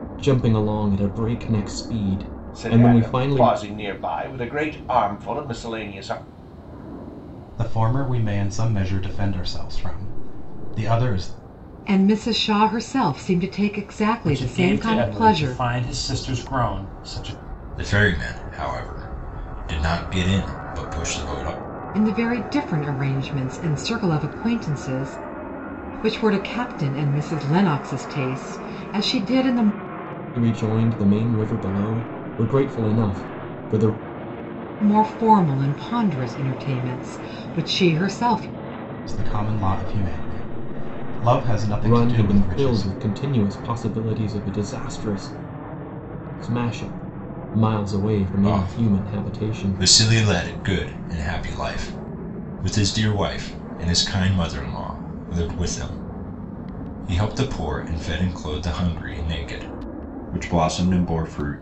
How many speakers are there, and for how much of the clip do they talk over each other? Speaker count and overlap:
6, about 8%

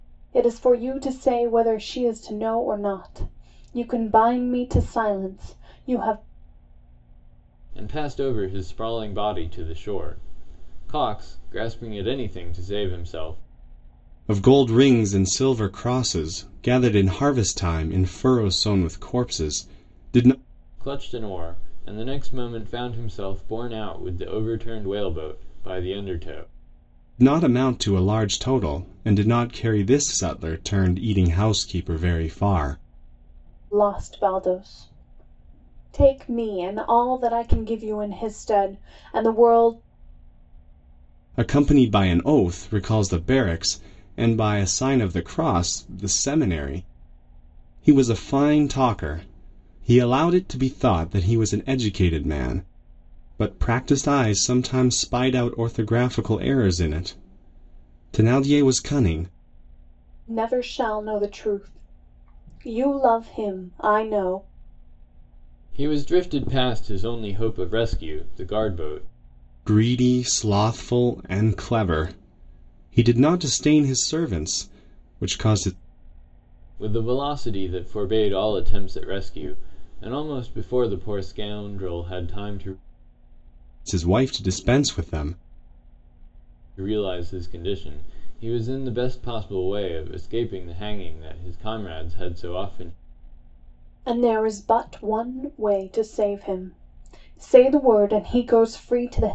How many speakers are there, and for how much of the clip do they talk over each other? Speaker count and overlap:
3, no overlap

